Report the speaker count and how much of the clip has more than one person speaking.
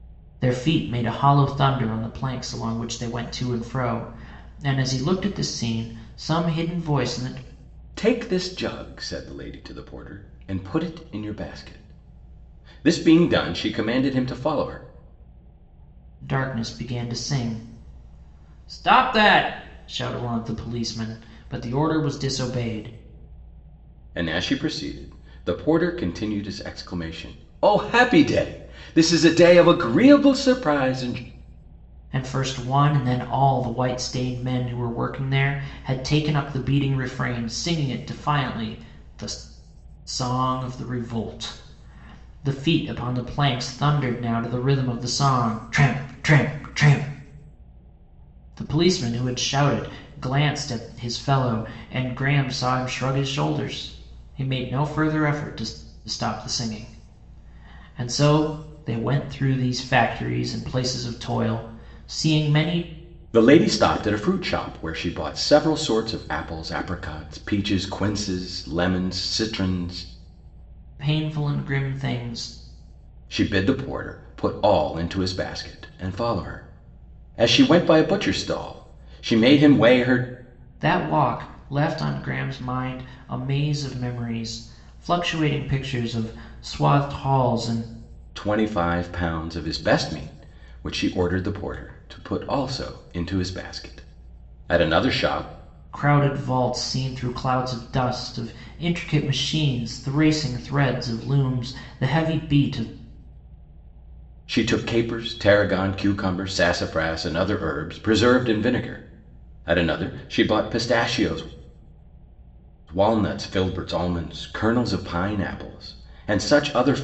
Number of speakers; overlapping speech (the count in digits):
2, no overlap